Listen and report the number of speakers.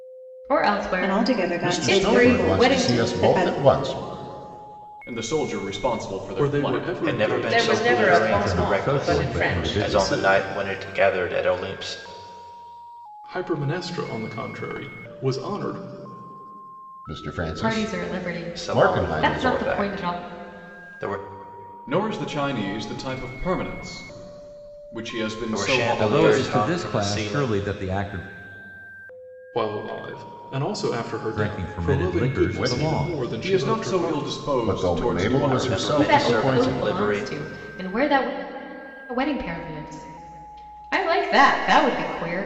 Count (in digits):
8